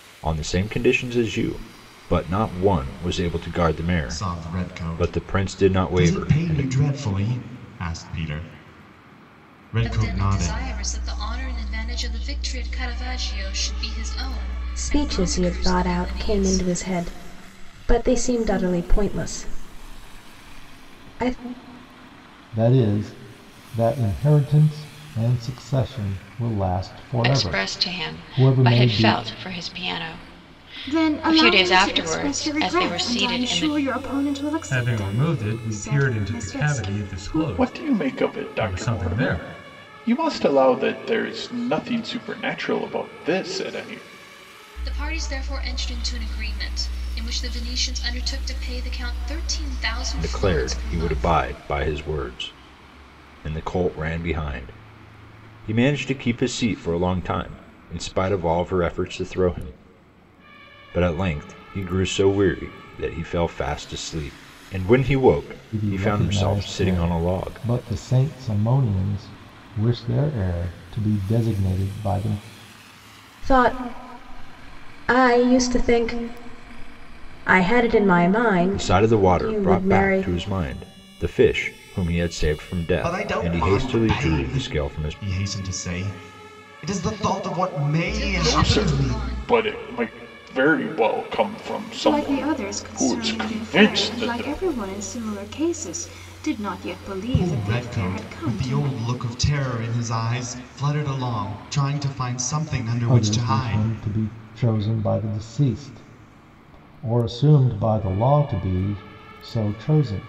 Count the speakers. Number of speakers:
9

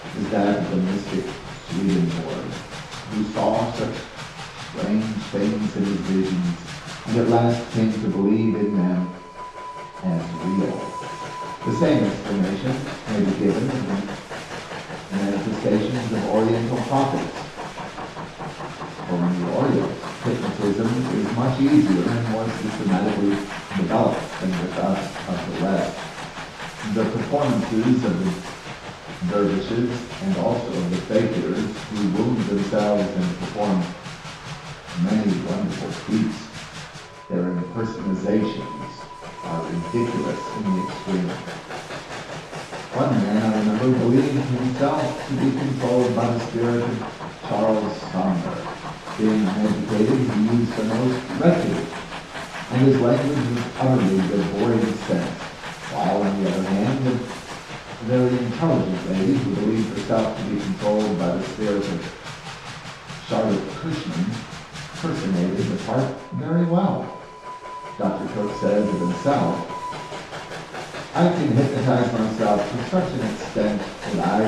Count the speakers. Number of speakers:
1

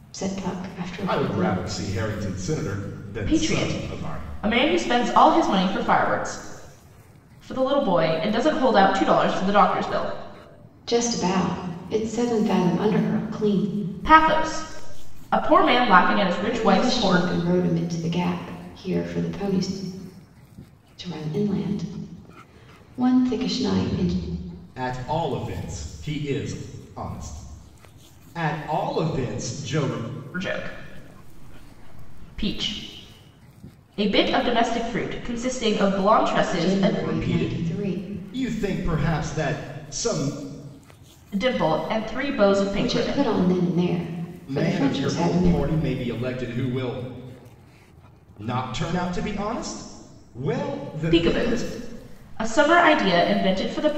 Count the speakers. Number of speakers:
3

